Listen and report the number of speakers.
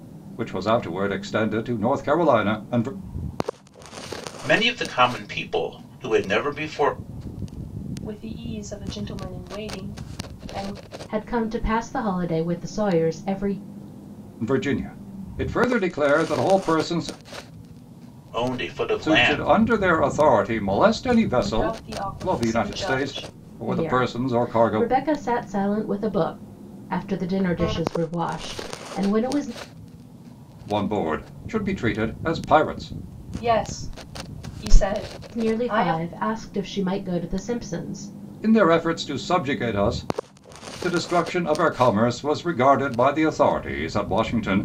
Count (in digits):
4